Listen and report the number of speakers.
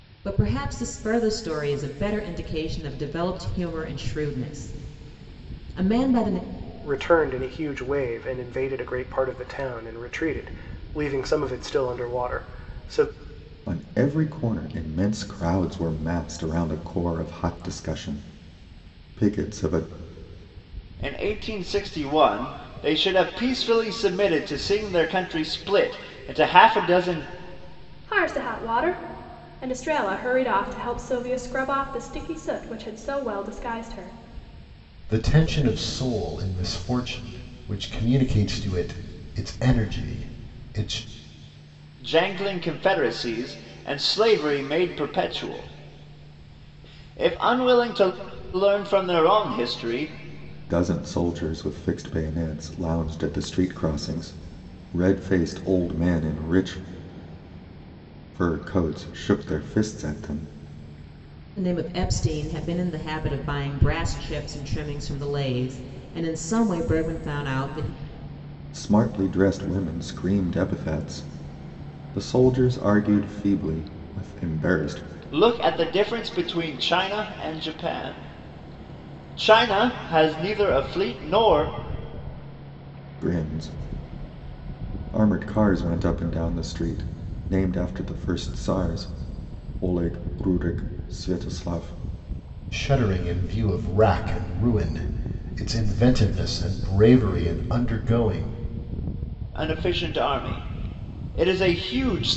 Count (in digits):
6